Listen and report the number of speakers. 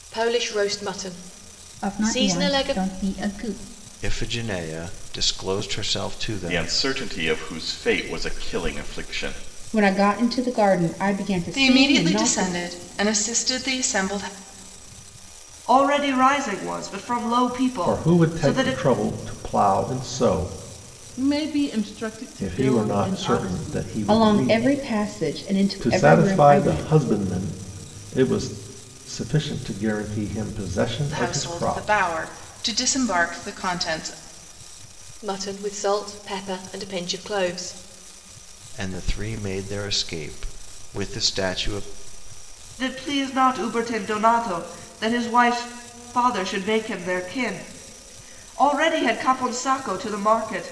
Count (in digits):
9